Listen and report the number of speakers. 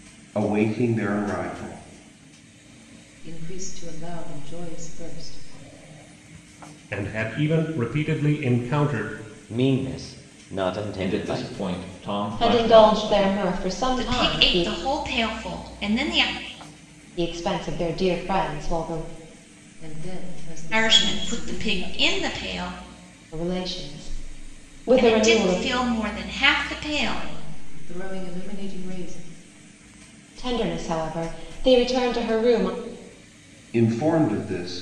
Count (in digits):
7